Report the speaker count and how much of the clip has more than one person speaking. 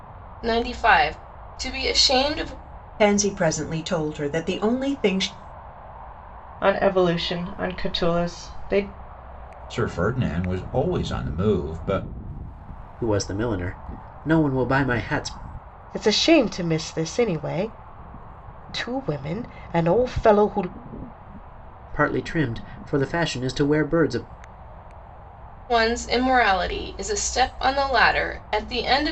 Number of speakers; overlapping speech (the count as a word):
six, no overlap